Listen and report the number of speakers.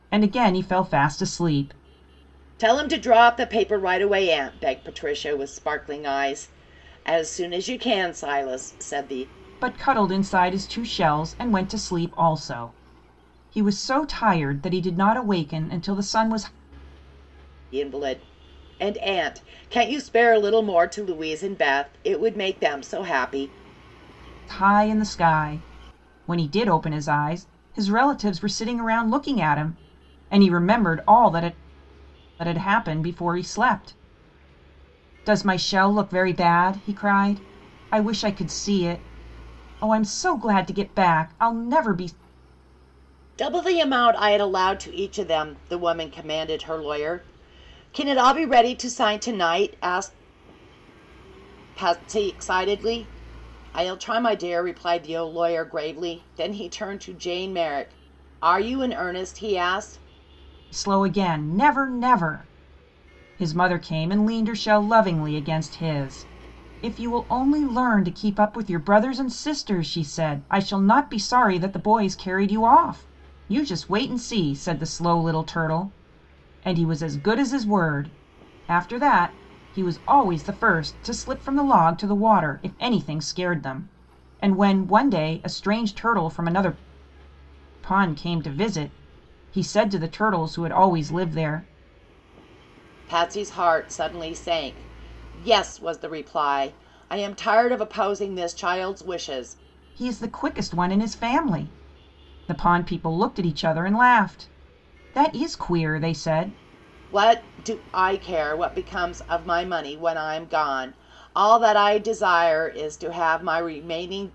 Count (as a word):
two